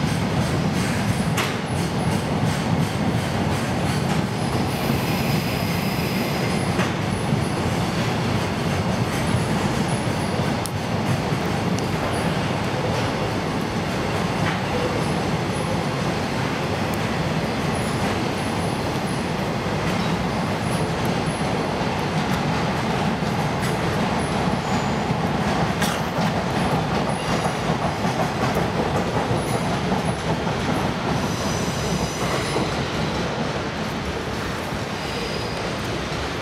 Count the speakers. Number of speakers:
zero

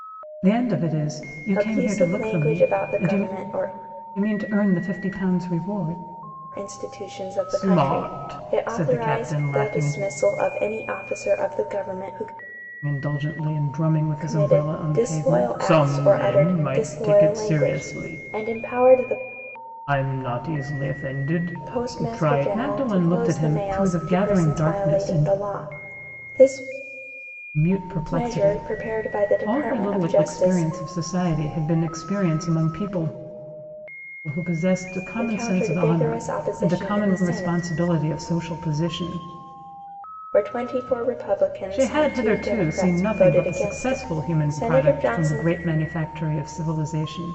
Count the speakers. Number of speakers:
two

